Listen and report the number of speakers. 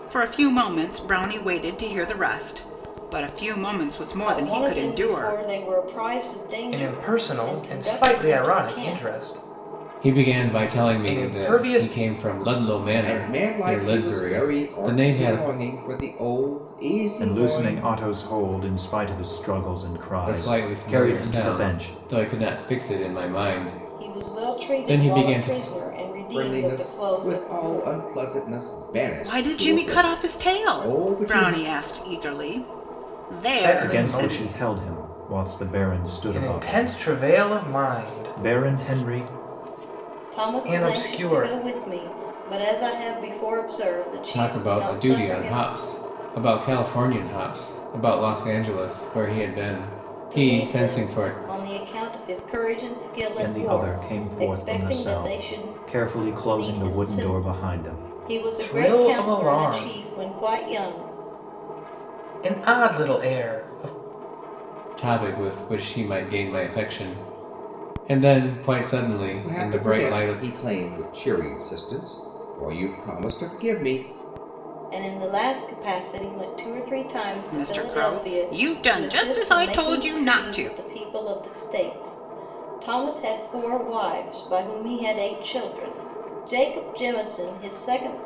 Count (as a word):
six